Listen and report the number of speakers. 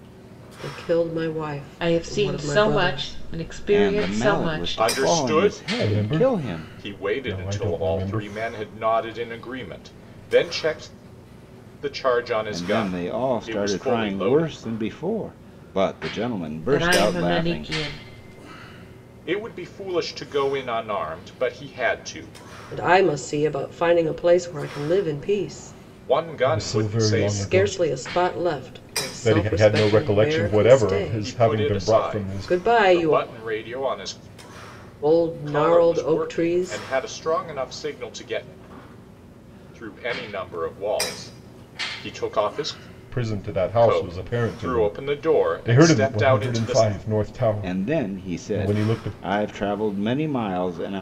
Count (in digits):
5